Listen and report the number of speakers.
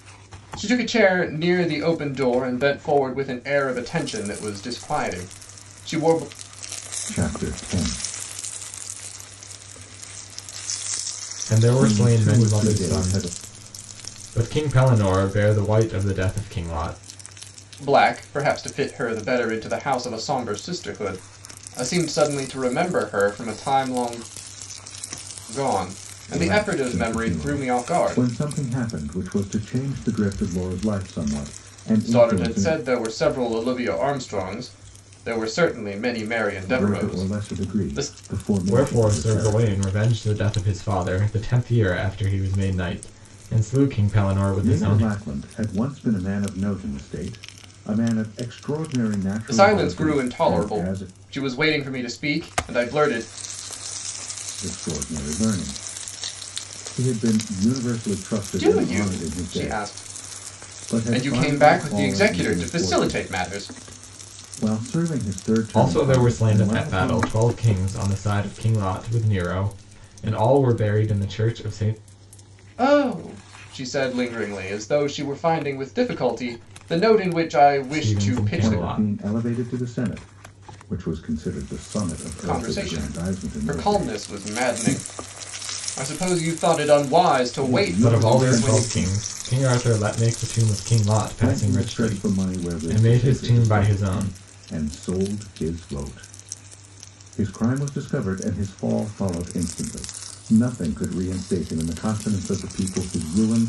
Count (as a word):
three